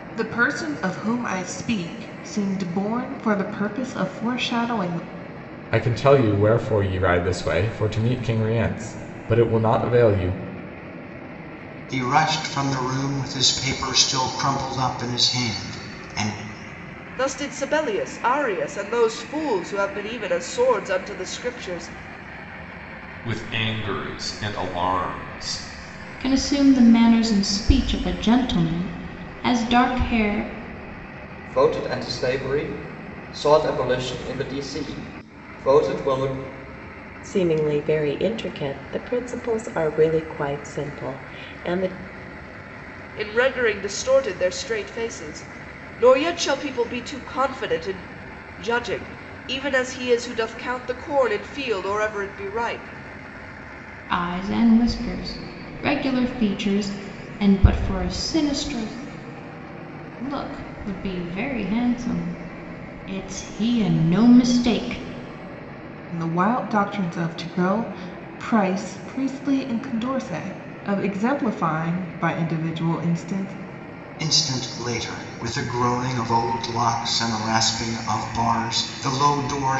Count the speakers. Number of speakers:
eight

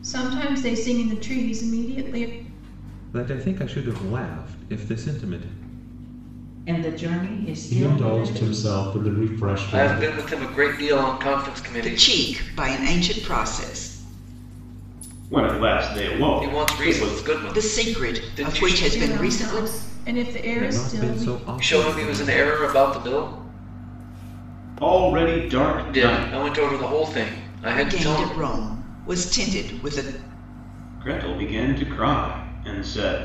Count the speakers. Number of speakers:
seven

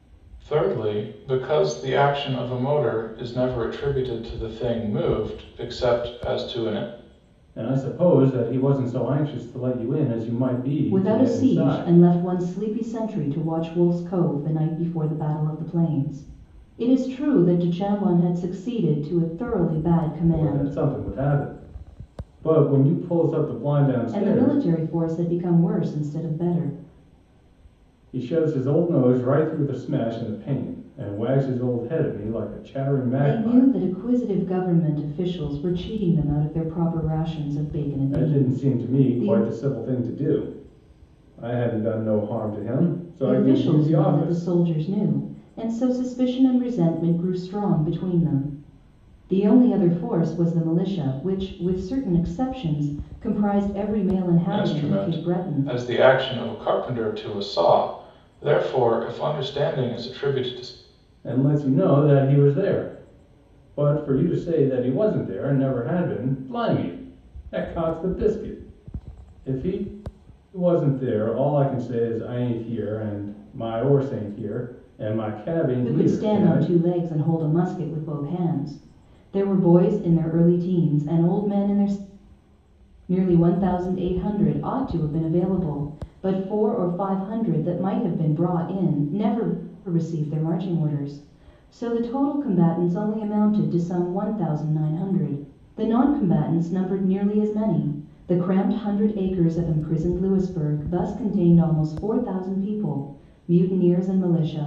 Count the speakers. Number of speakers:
three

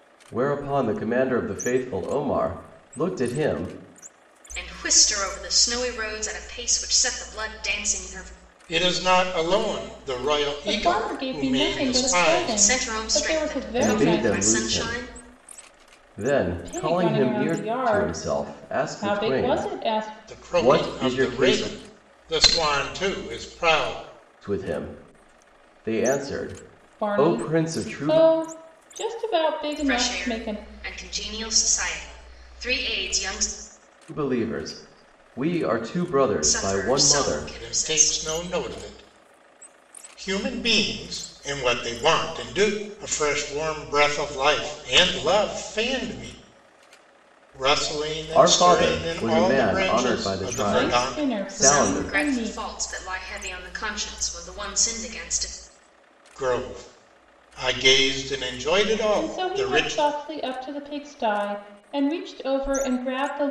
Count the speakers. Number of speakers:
four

